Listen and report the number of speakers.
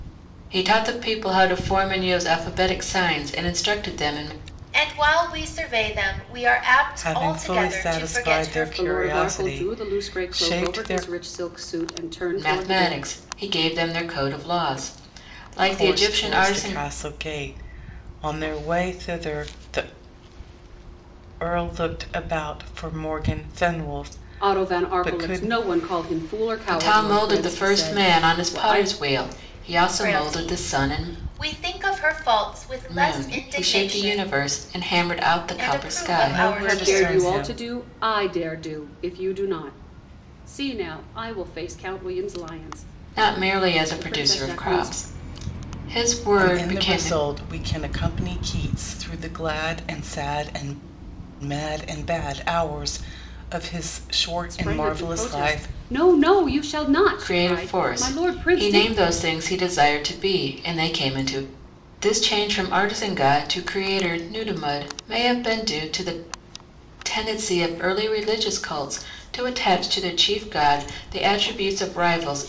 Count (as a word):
four